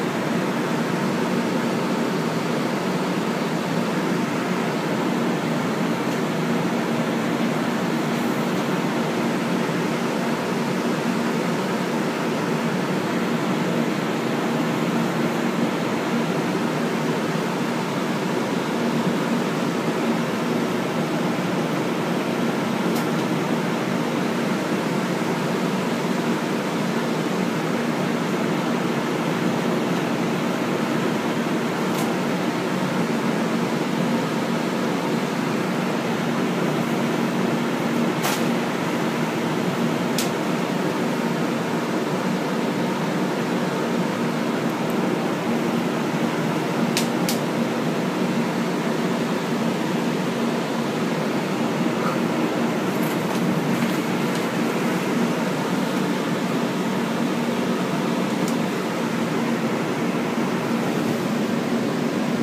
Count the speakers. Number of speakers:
zero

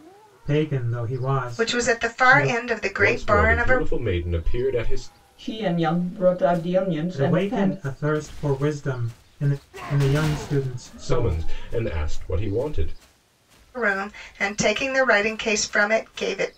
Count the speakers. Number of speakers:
four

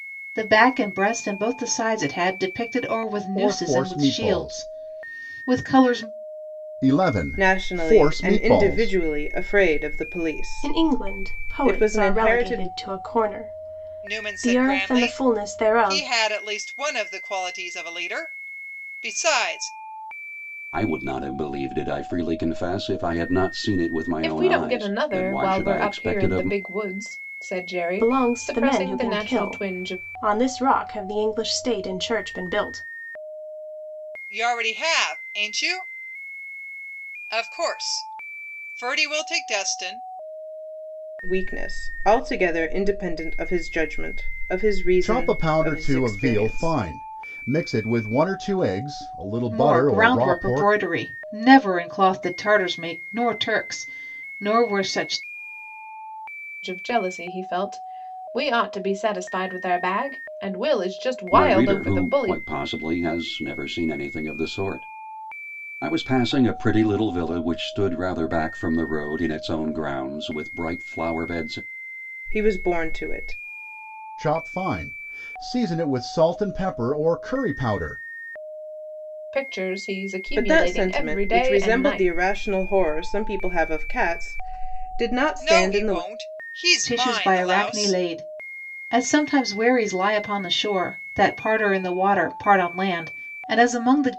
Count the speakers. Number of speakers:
seven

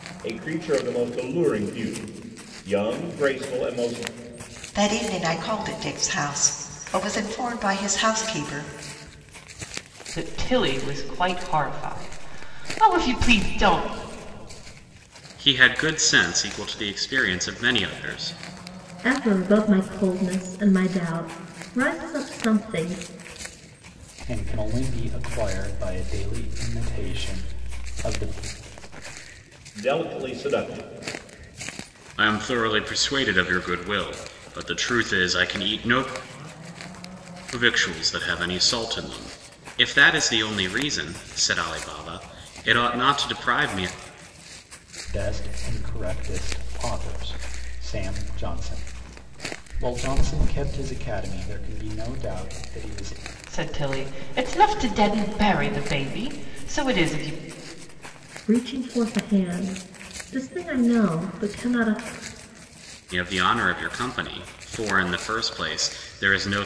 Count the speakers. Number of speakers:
six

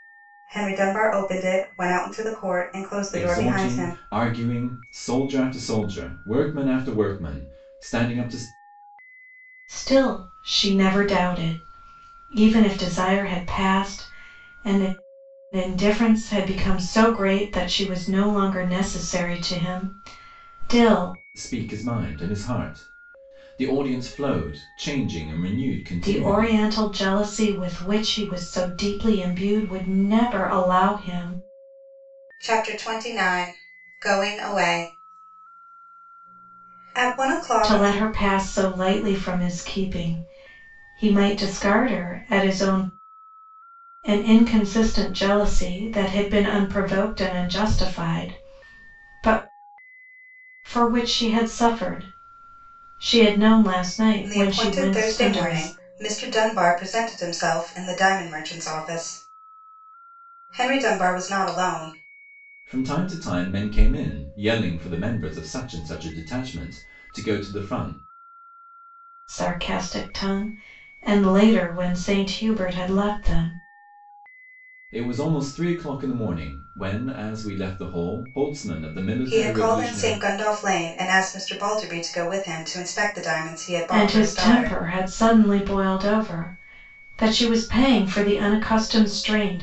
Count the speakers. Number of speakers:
three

